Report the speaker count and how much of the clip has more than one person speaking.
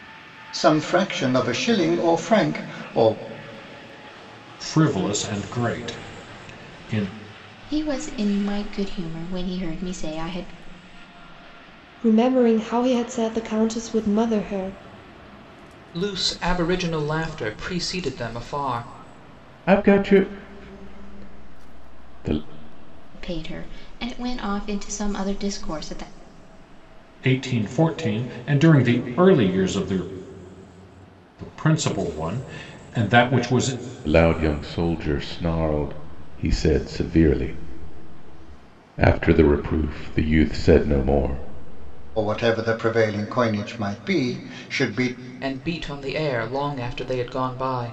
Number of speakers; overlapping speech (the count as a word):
six, no overlap